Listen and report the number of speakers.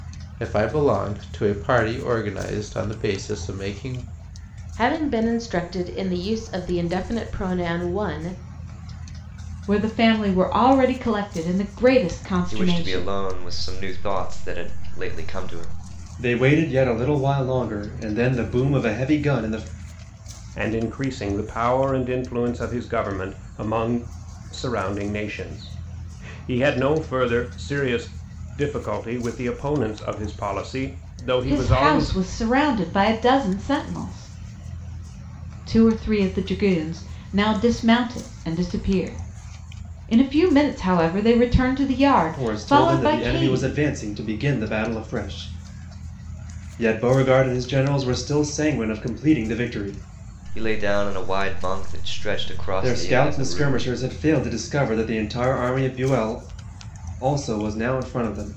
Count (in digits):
6